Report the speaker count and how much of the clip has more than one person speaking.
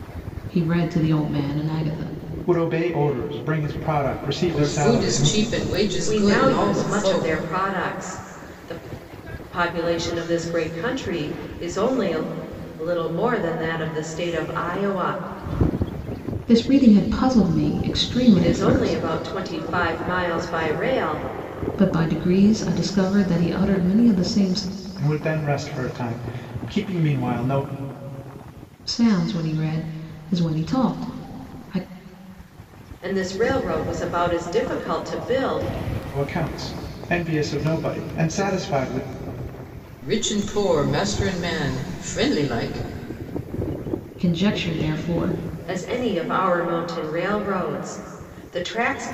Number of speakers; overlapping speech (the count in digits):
4, about 6%